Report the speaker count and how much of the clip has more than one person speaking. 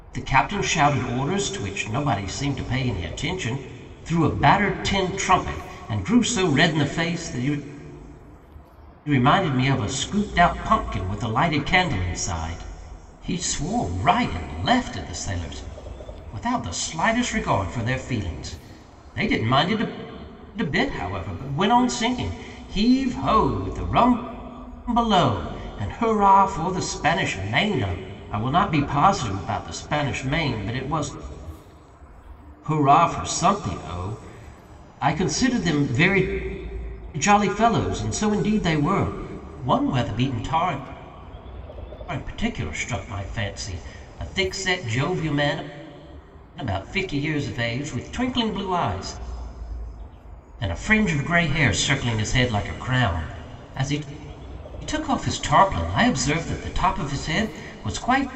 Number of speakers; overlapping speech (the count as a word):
one, no overlap